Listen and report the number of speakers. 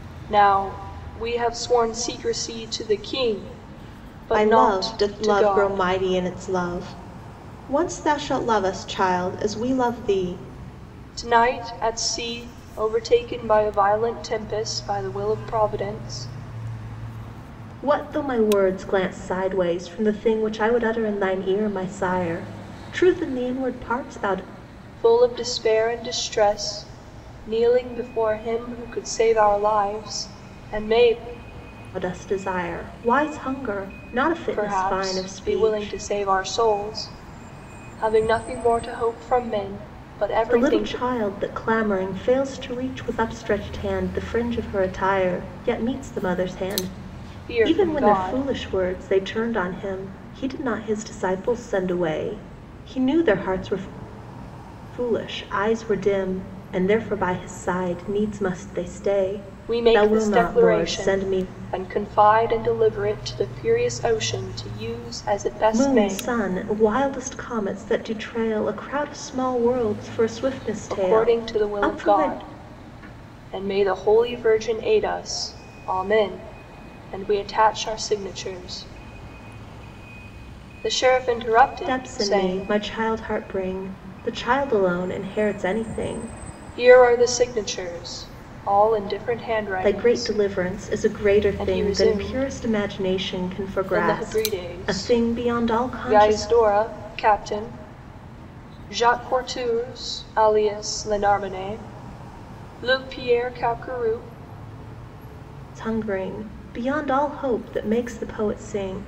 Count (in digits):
2